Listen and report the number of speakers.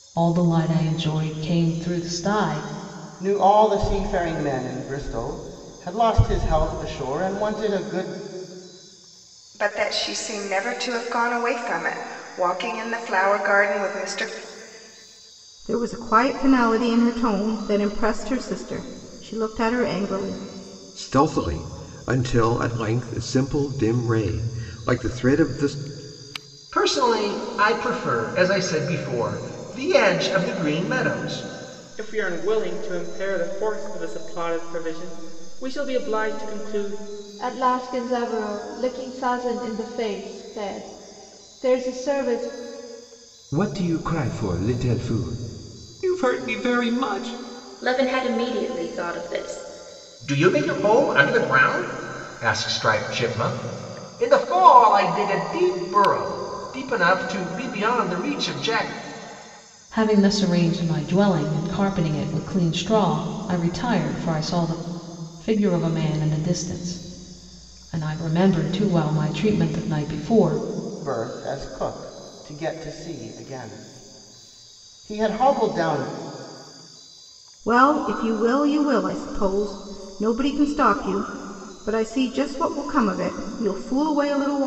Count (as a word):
ten